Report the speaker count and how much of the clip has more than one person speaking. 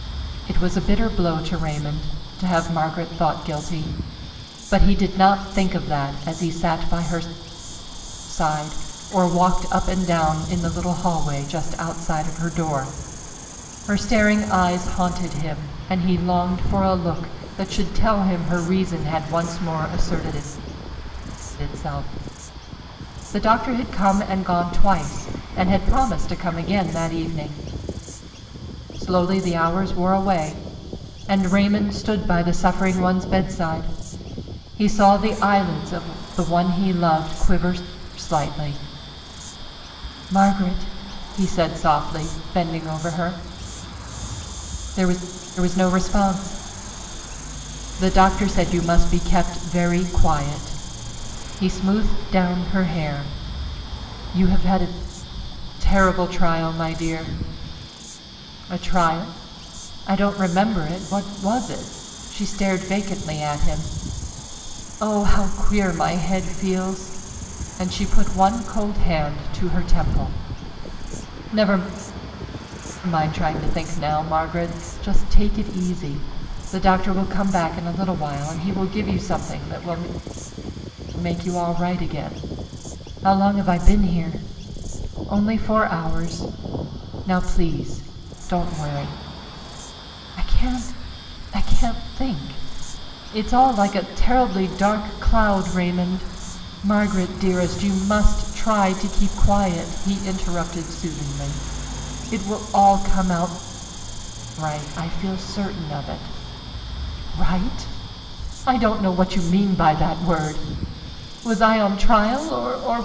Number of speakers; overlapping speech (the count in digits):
1, no overlap